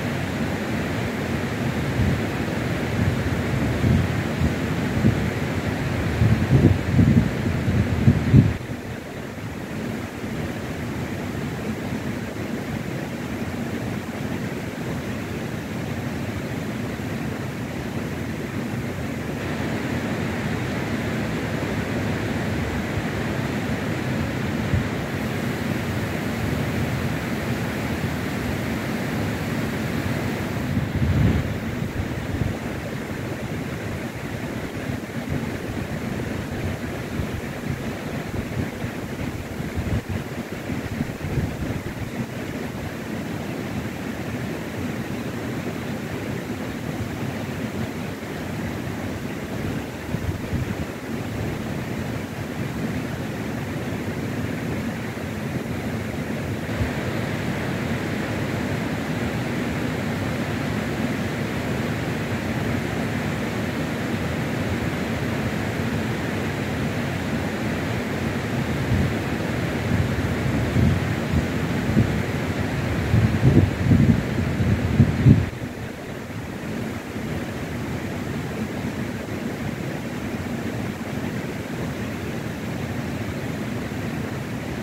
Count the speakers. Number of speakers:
0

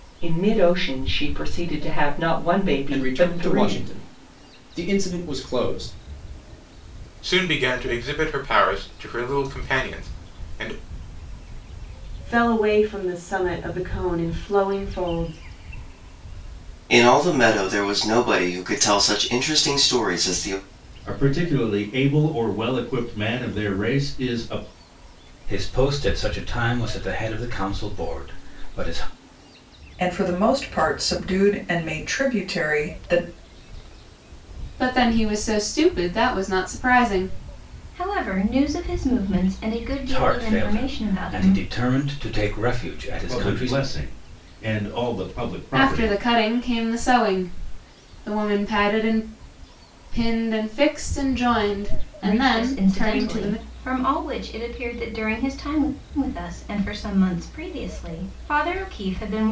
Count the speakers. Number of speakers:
10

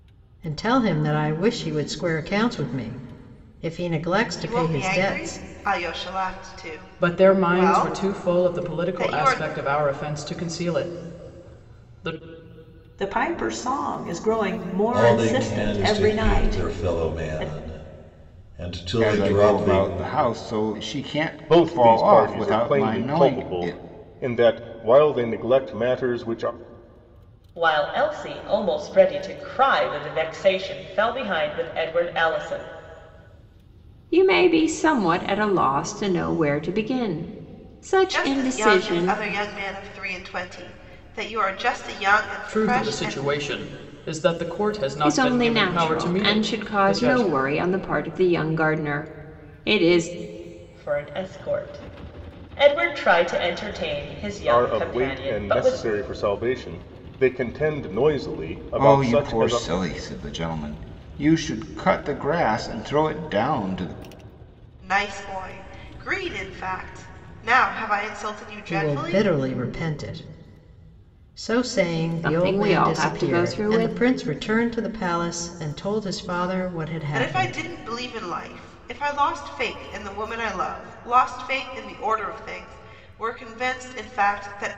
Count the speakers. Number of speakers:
9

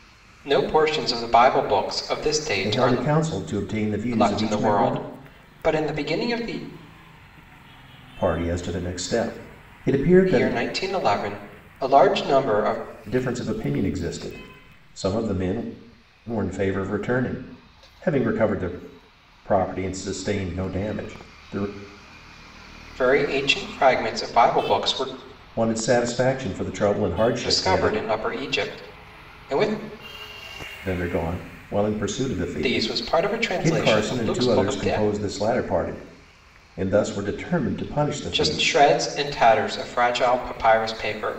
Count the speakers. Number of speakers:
2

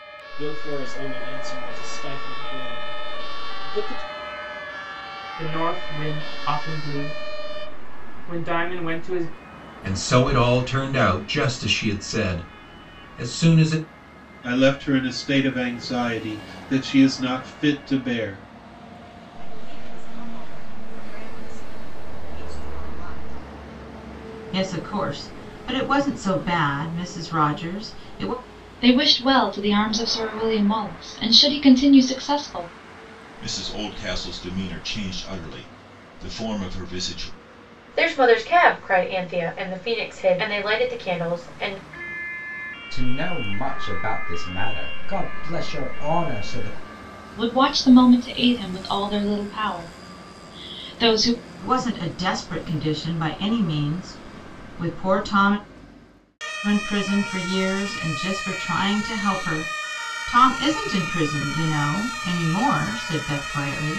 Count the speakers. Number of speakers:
10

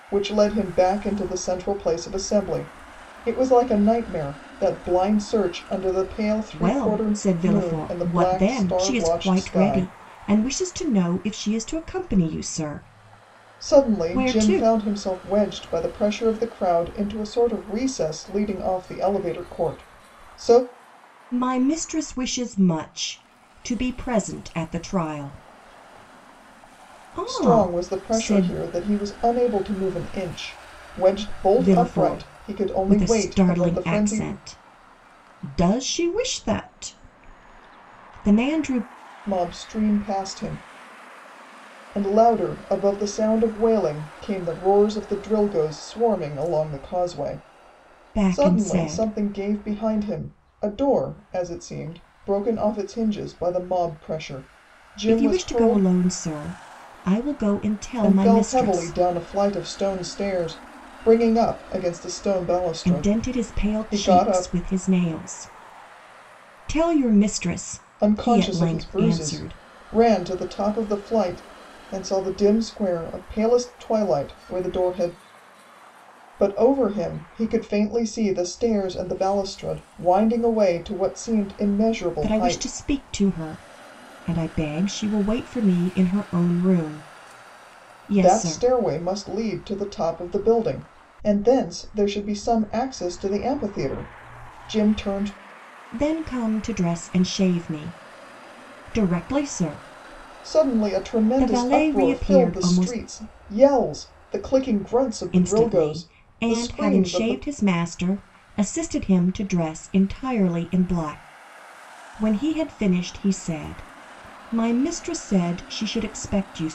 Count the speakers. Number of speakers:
2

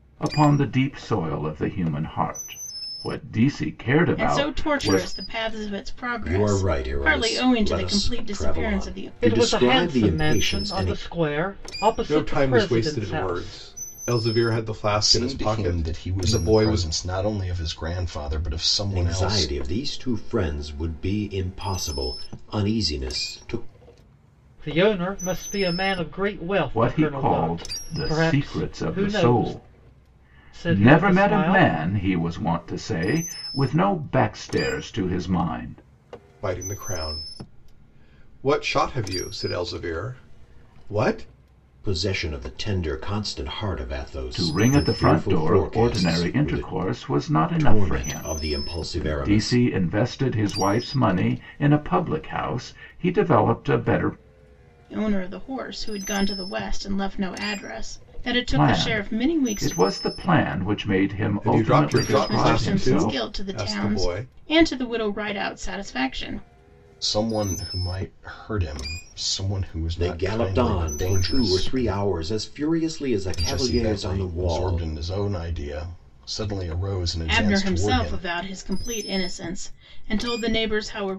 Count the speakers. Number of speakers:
6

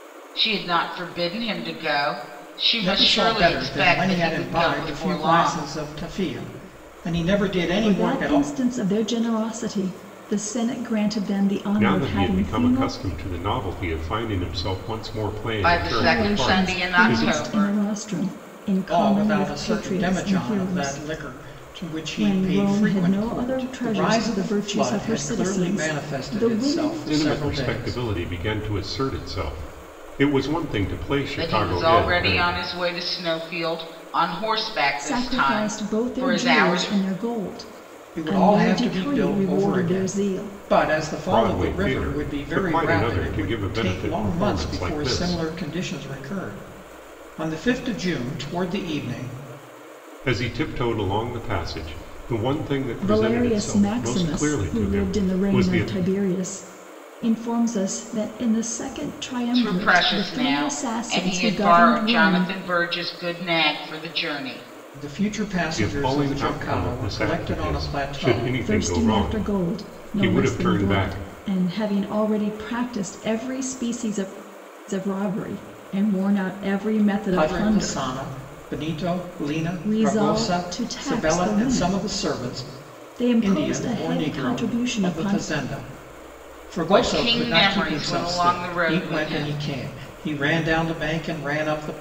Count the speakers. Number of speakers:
4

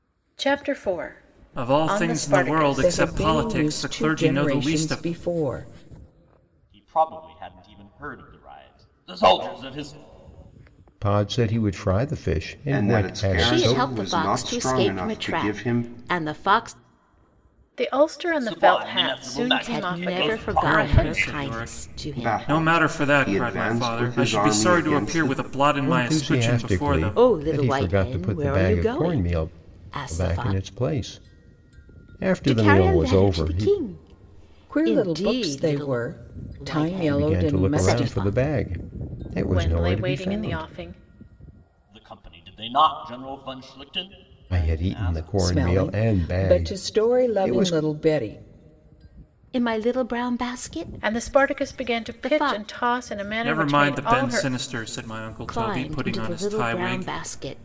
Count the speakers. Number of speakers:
7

